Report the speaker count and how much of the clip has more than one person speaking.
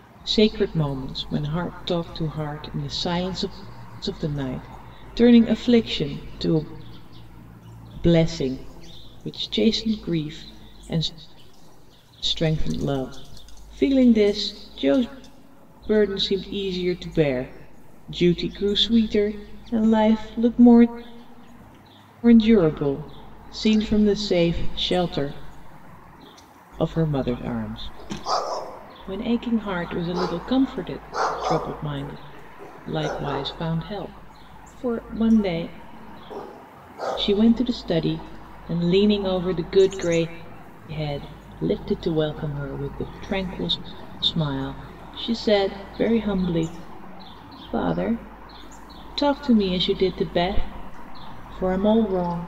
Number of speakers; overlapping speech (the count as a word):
one, no overlap